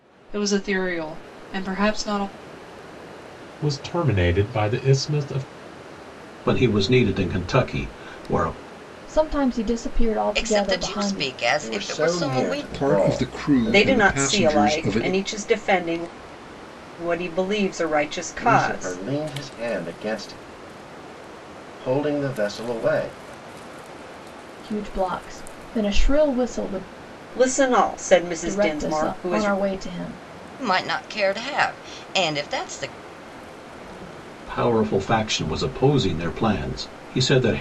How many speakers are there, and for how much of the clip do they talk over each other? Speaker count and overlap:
eight, about 17%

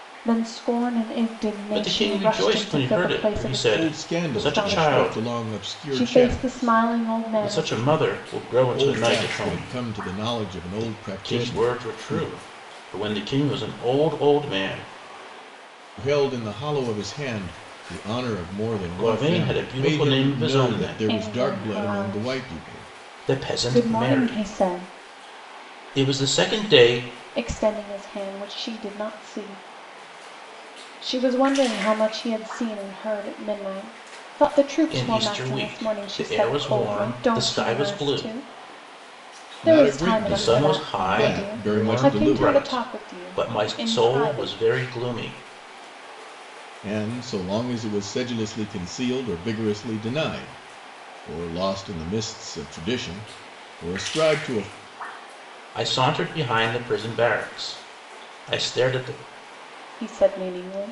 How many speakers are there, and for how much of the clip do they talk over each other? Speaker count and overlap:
three, about 38%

